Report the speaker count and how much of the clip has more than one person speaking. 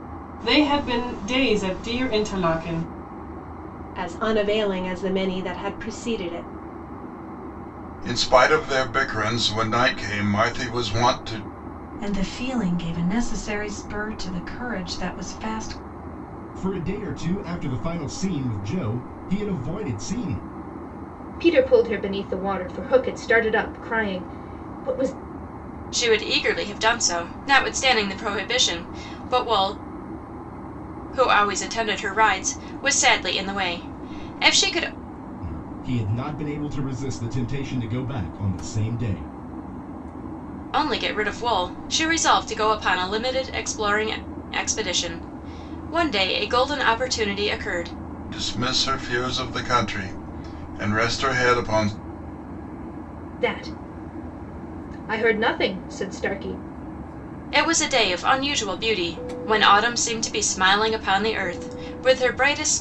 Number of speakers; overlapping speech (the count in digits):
7, no overlap